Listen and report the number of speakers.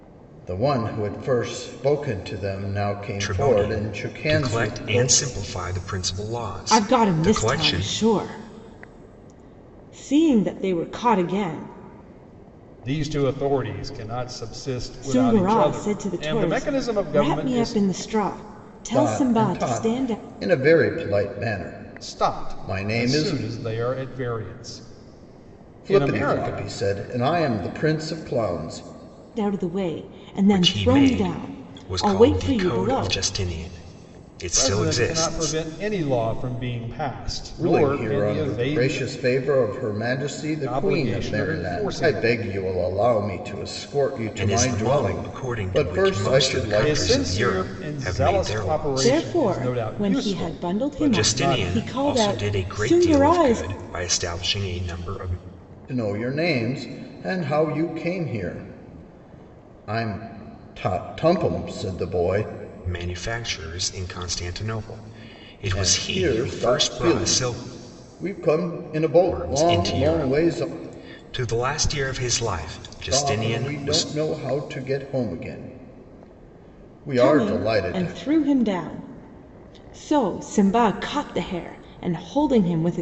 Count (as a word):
four